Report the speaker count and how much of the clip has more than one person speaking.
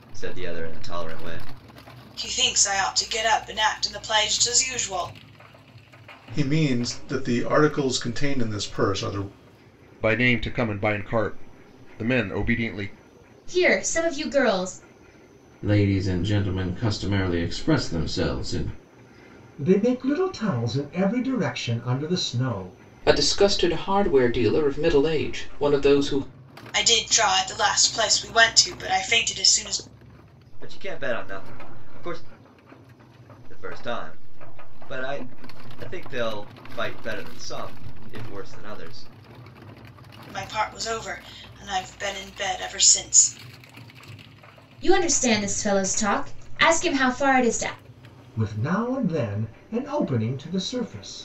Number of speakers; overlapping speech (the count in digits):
8, no overlap